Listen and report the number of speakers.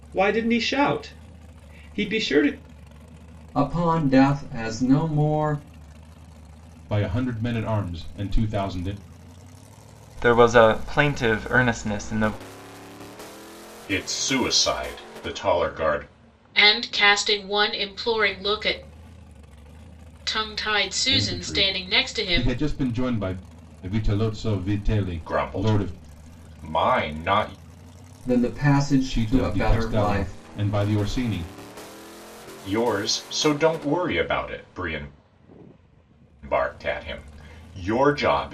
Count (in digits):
6